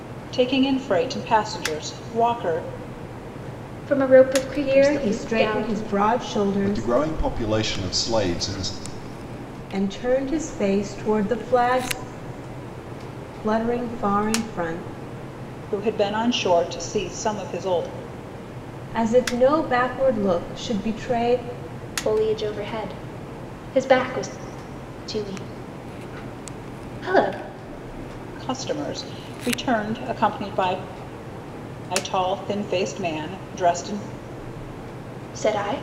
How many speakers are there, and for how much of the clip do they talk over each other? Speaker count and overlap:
four, about 5%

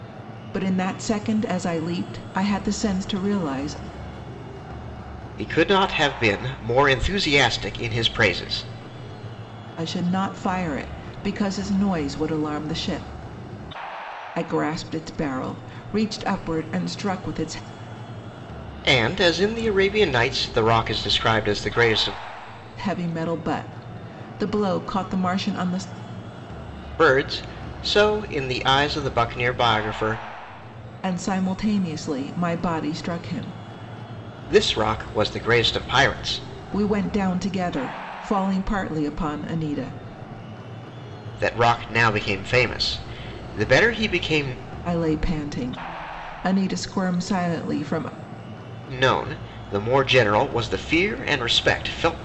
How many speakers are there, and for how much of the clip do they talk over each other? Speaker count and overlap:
two, no overlap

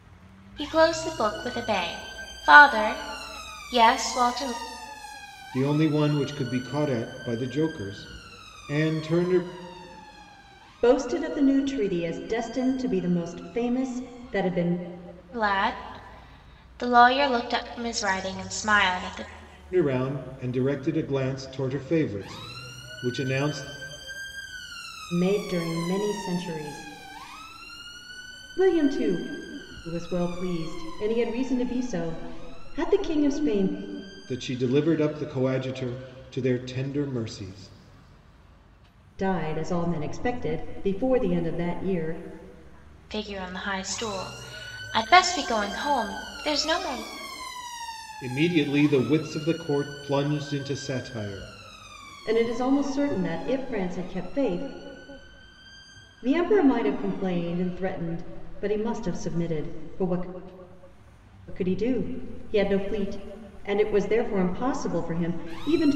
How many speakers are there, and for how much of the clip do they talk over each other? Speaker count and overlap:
three, no overlap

